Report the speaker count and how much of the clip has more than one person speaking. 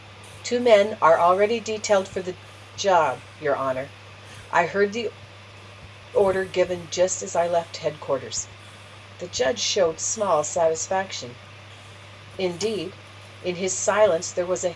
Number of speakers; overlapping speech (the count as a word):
one, no overlap